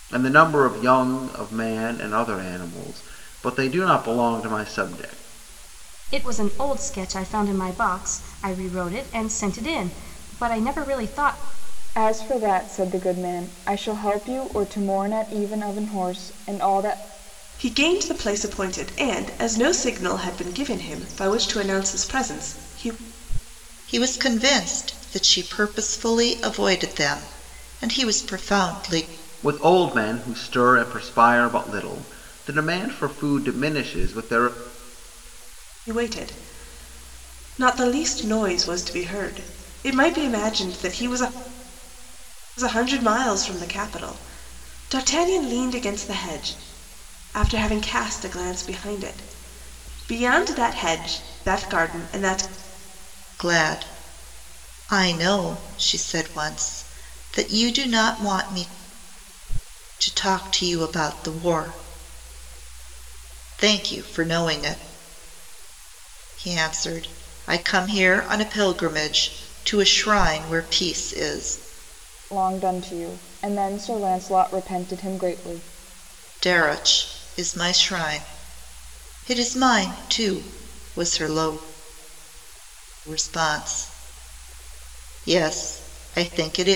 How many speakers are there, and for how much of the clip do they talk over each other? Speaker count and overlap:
five, no overlap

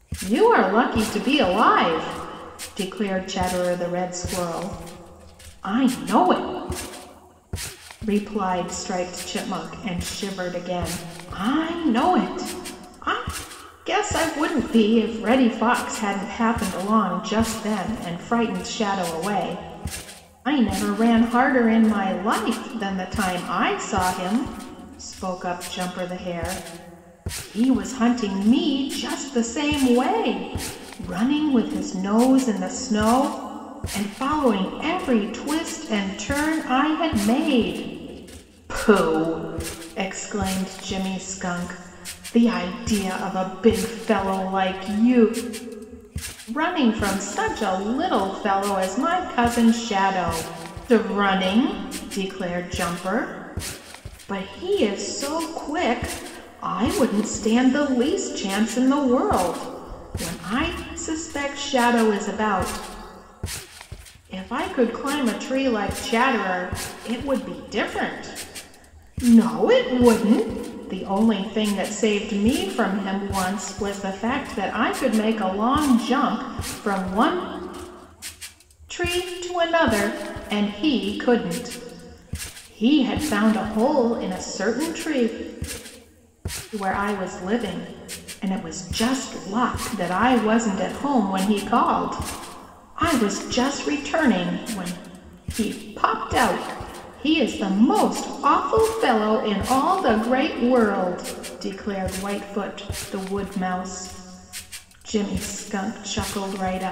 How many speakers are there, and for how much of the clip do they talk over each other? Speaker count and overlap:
one, no overlap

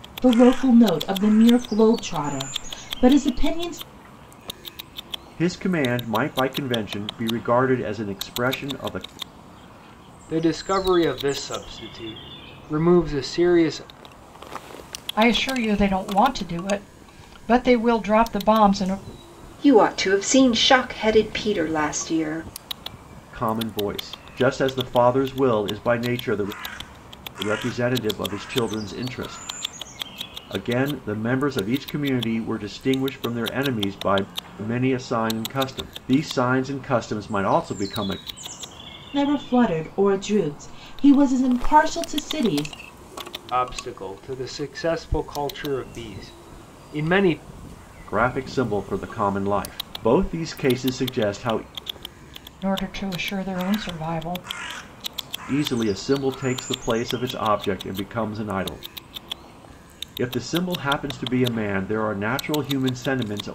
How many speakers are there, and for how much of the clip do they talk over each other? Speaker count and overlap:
five, no overlap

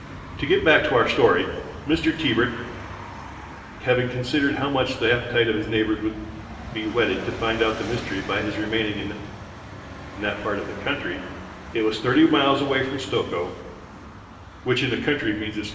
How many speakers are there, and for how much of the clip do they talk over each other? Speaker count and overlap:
one, no overlap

